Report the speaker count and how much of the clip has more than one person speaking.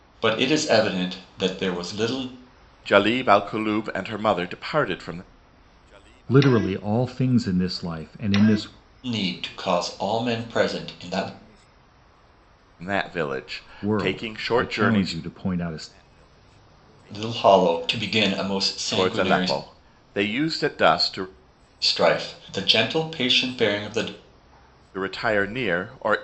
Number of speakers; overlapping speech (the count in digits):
3, about 8%